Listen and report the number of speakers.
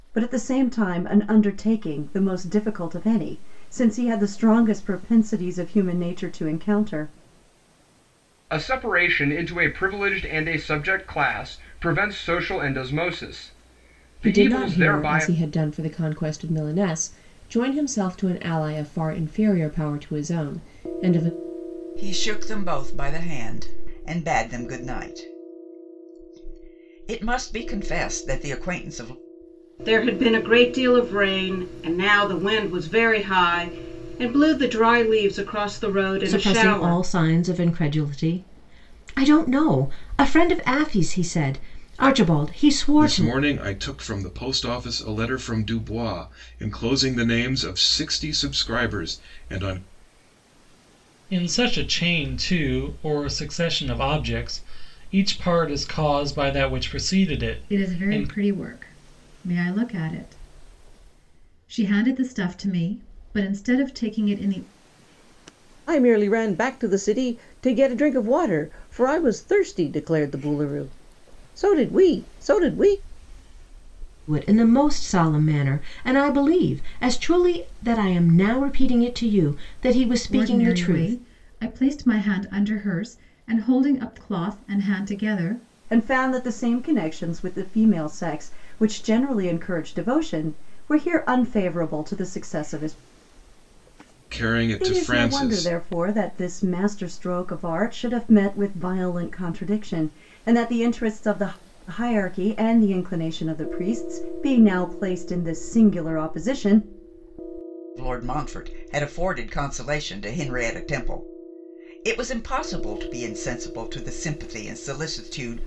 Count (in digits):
10